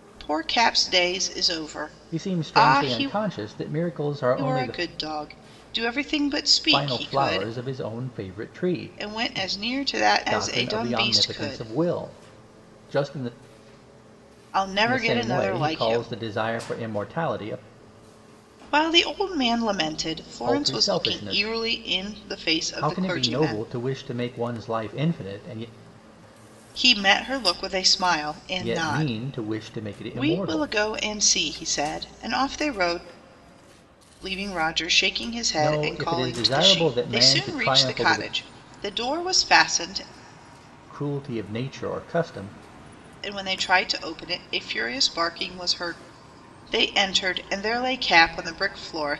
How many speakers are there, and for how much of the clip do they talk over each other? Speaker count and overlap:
2, about 24%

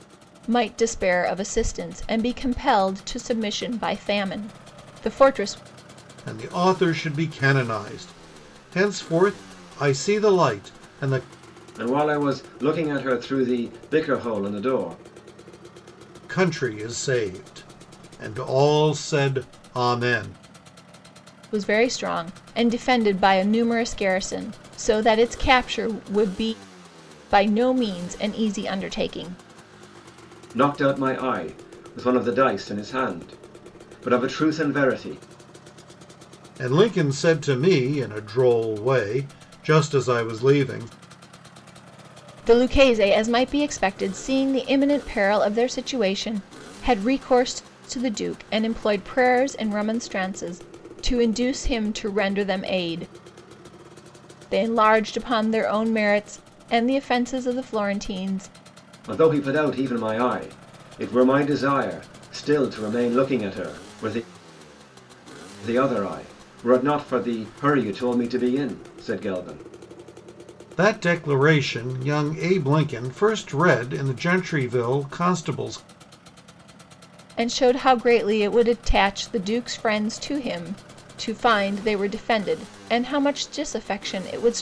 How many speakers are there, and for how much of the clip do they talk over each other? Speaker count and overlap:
3, no overlap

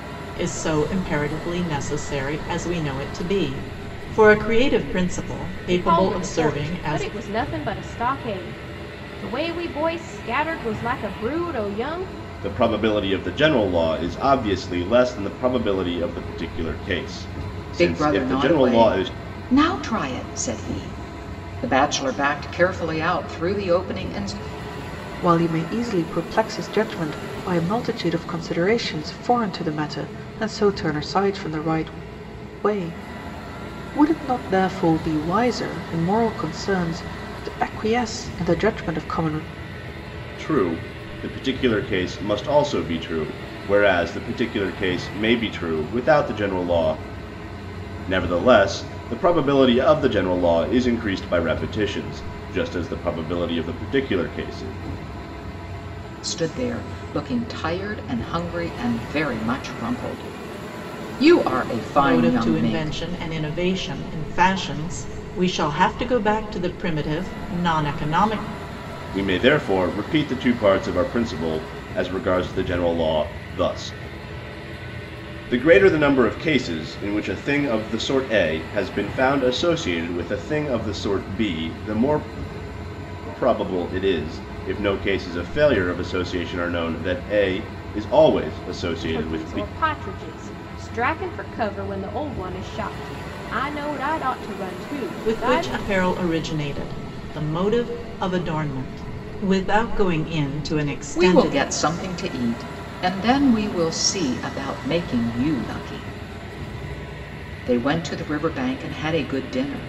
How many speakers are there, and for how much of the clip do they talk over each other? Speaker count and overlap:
5, about 5%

